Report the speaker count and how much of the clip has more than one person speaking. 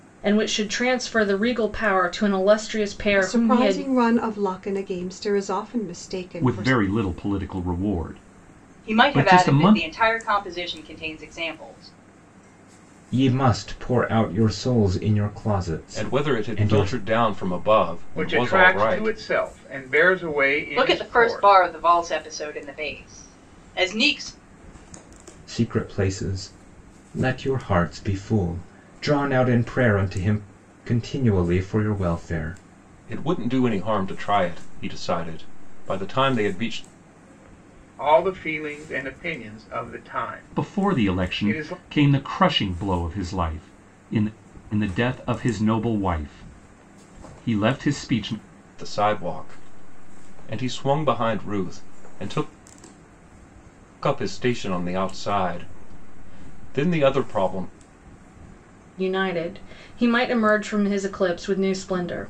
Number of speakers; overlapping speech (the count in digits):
7, about 11%